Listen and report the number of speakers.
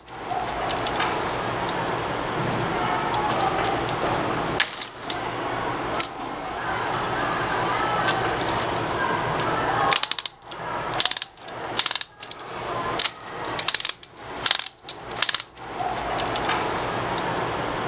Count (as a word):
zero